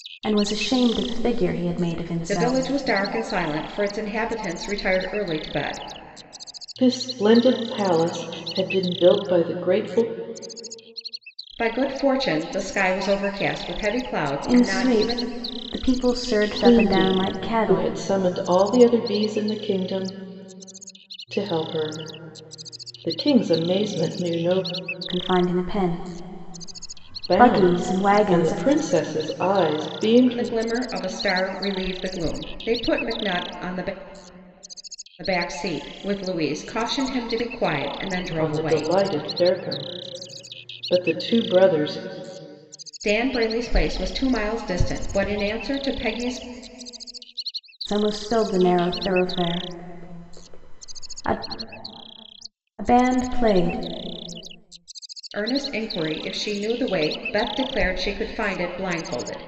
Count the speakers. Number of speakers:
3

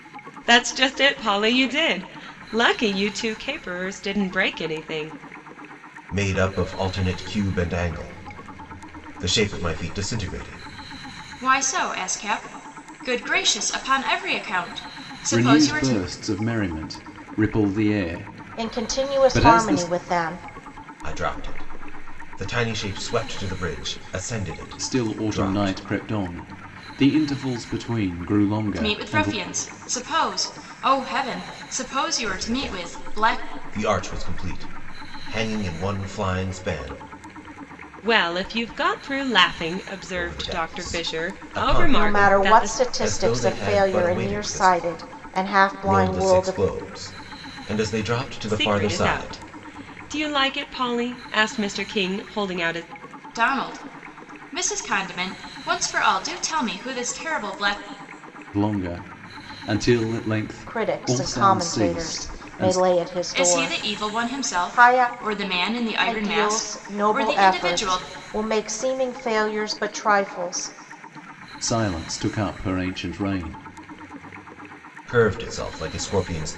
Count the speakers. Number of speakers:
5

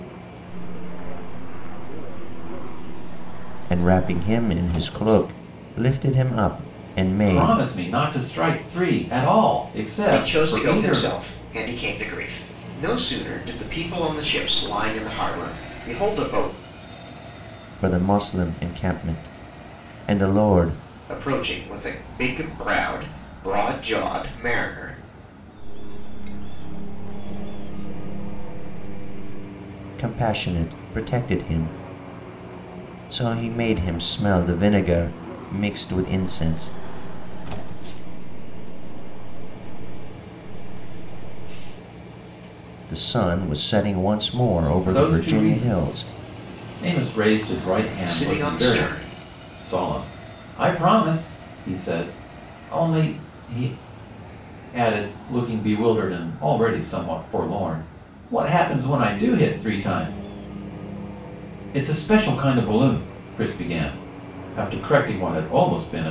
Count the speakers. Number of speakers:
4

